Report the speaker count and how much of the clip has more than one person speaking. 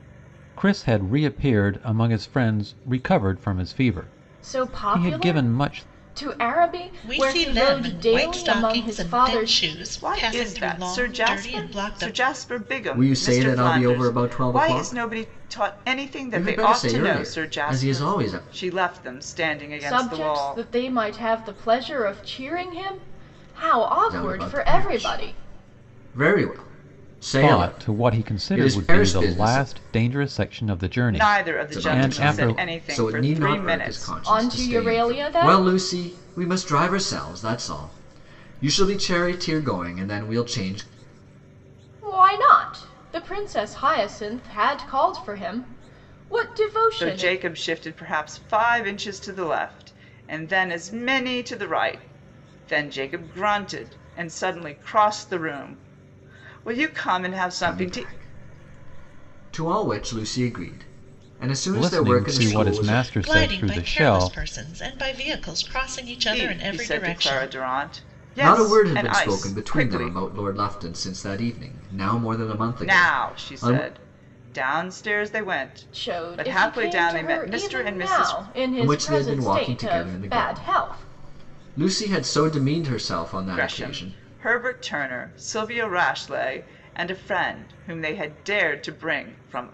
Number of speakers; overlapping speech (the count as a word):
five, about 38%